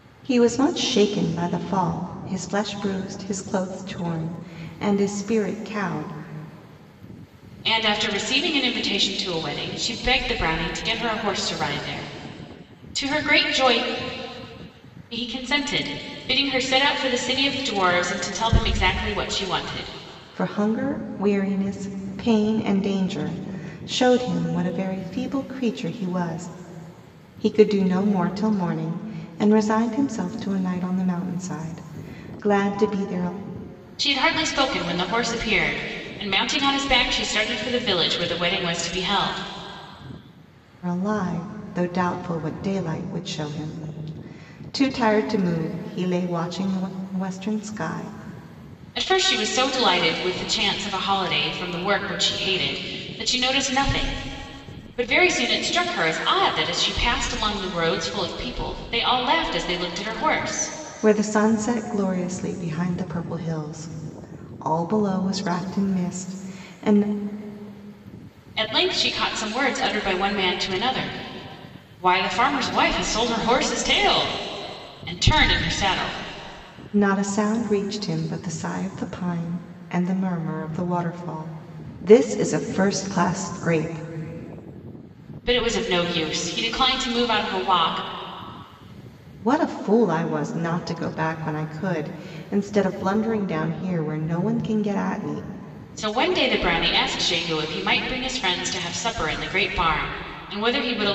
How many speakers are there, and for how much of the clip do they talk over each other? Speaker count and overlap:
2, no overlap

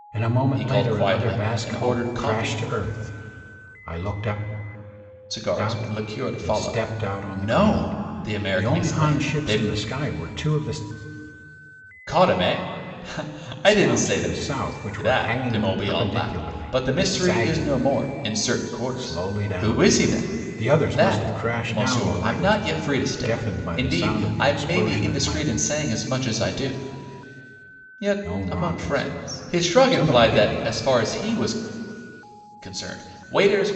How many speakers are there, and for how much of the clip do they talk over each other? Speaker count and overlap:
2, about 49%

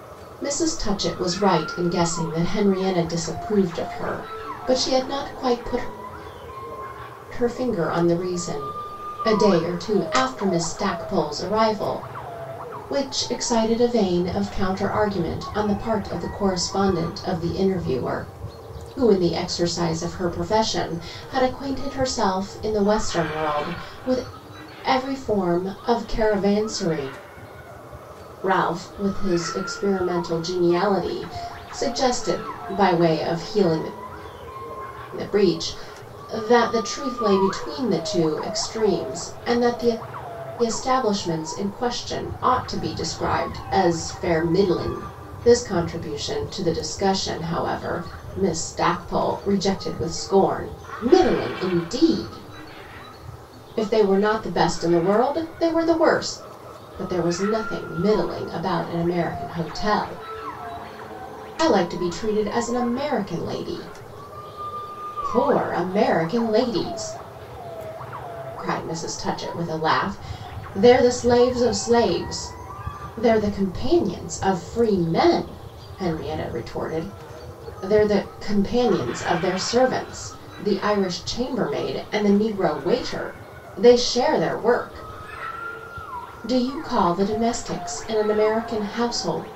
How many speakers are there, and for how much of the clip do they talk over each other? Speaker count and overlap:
1, no overlap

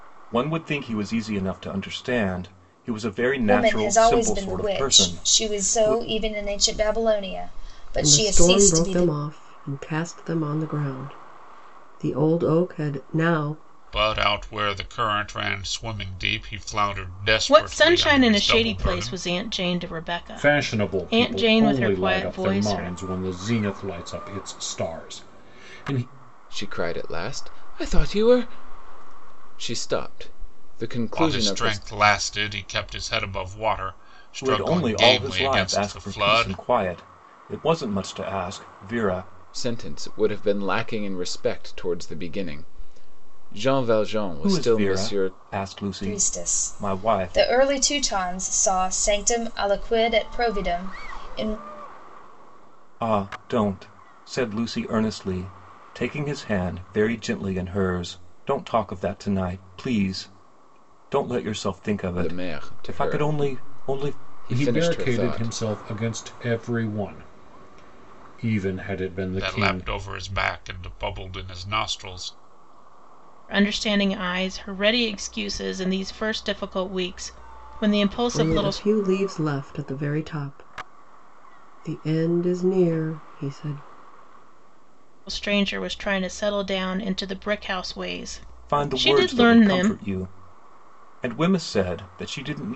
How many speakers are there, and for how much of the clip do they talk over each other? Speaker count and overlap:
7, about 21%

